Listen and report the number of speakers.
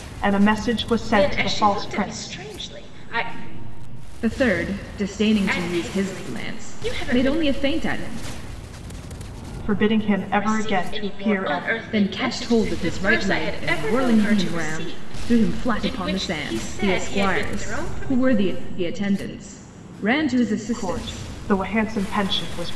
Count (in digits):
3